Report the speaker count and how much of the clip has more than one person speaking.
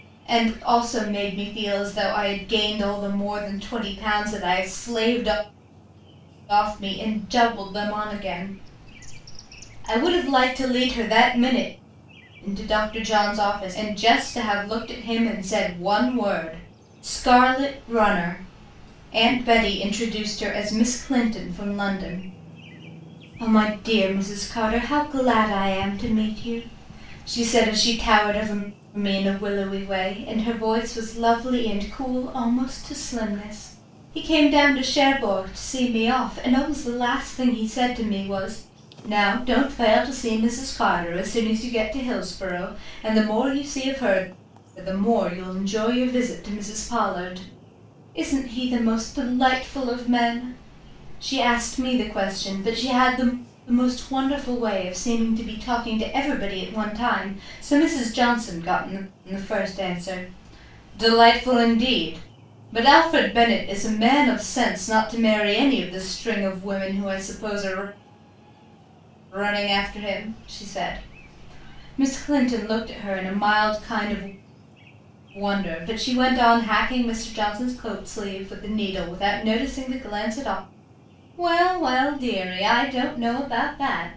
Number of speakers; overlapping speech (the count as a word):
one, no overlap